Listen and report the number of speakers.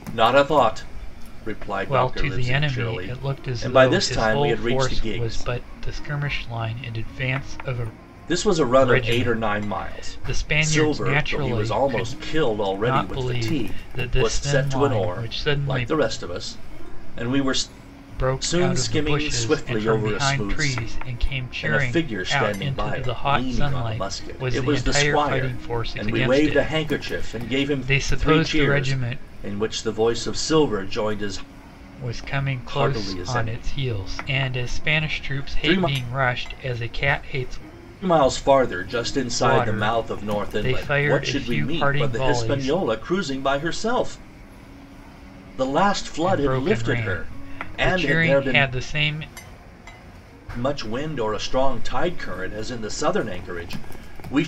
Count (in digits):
2